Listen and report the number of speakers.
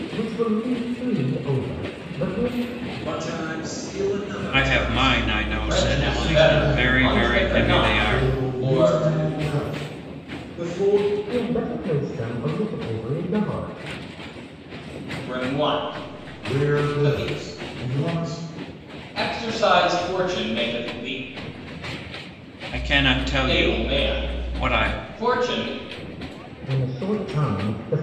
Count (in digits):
5